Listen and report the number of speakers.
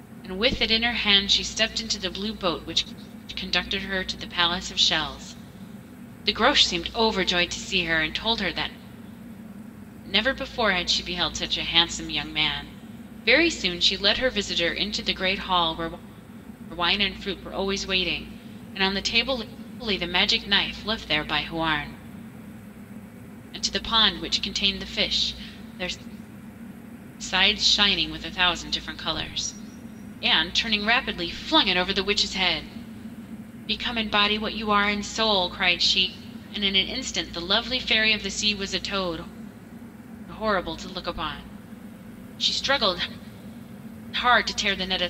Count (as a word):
one